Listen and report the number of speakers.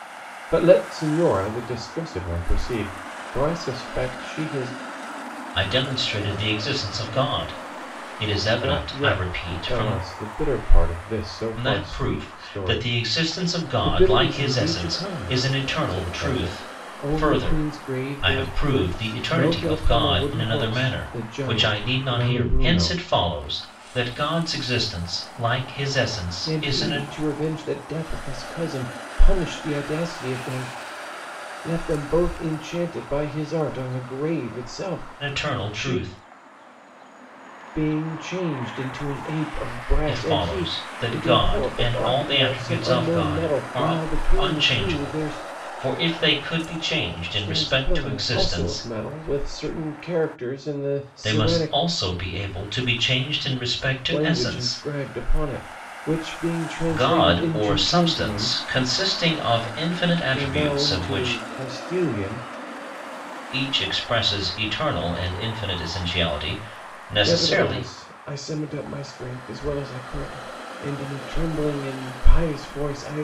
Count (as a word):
two